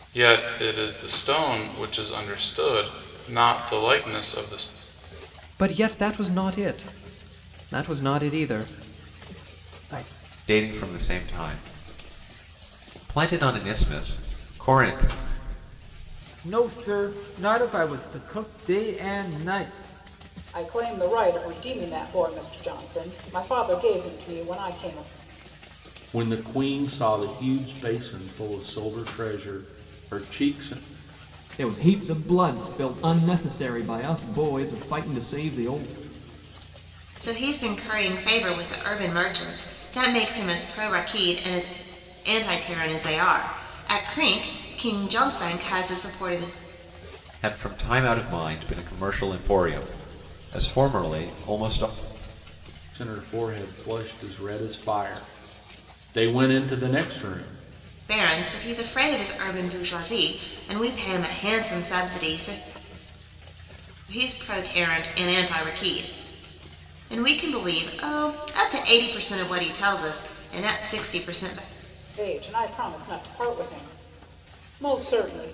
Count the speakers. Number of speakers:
8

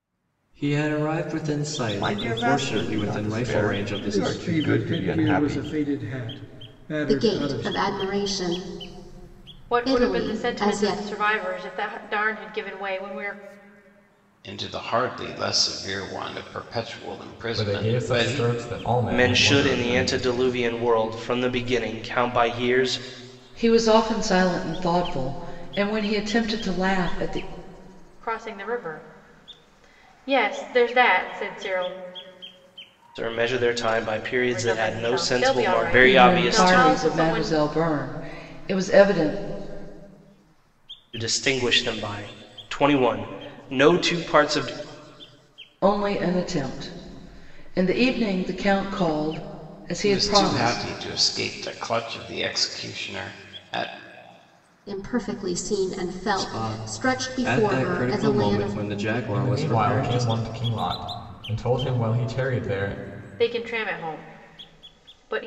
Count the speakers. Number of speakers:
9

